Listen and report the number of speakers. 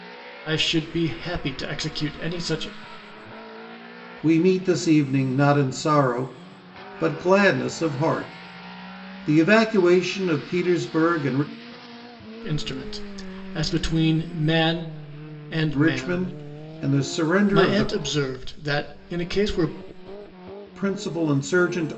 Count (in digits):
2